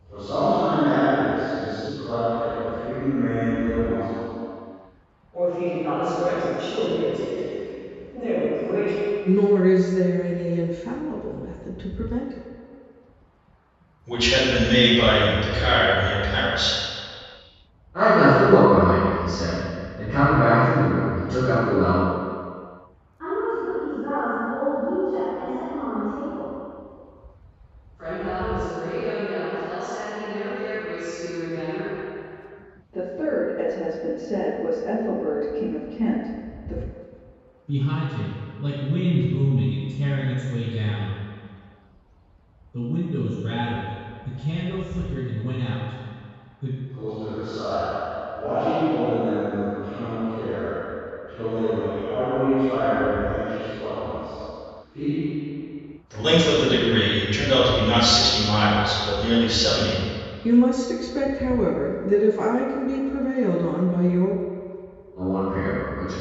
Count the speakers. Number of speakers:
nine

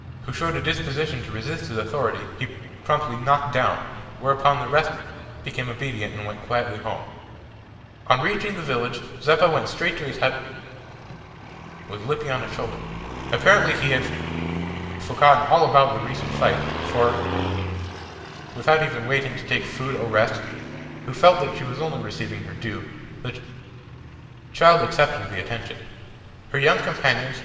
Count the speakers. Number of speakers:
one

